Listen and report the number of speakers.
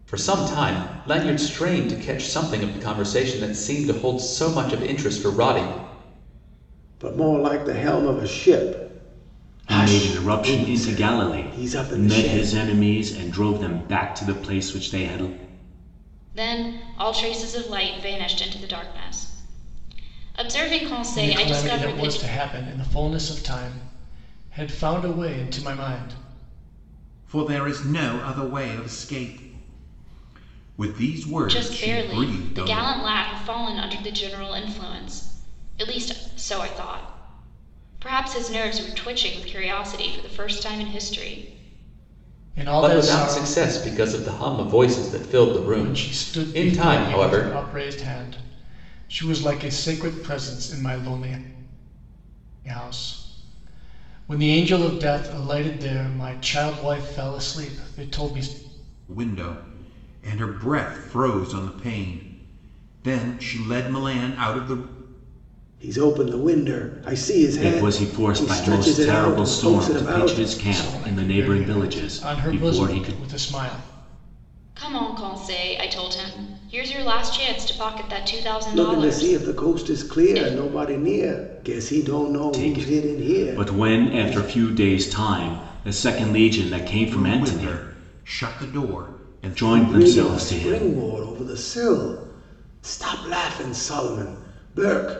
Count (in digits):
6